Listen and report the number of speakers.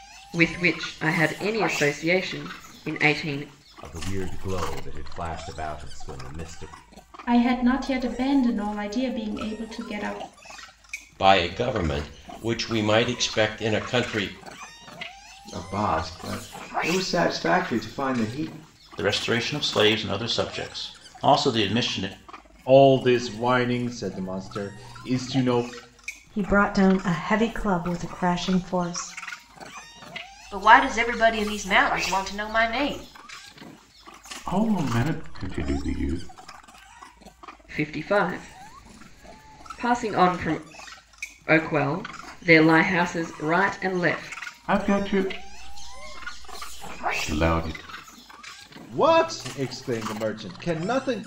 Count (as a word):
ten